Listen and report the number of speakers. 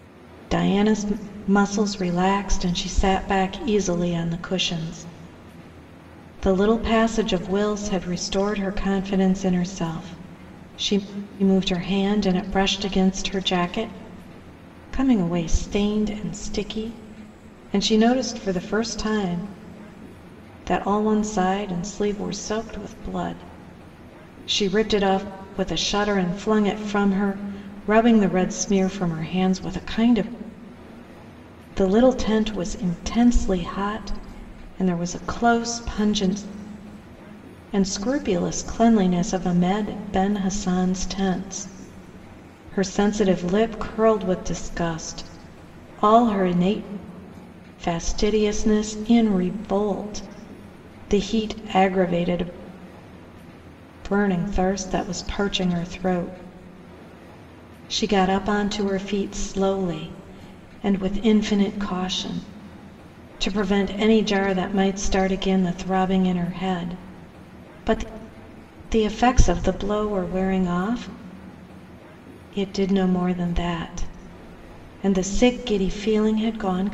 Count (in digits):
1